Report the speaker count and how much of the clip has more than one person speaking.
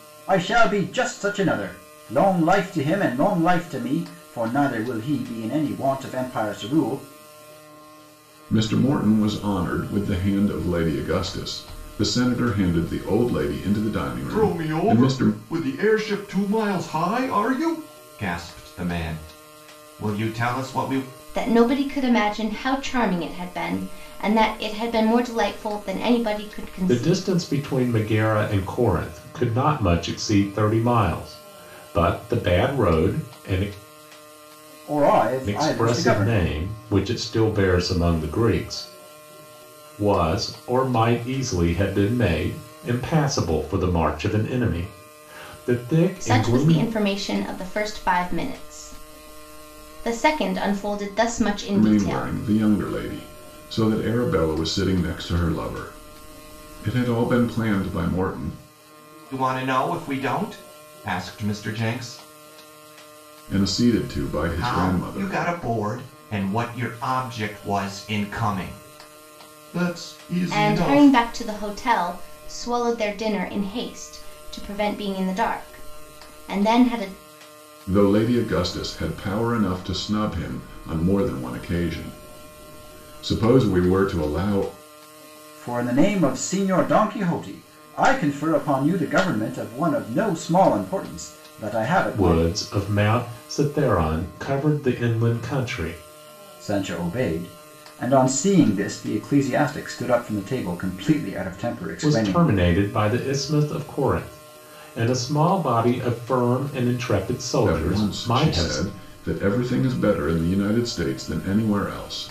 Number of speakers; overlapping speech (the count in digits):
5, about 7%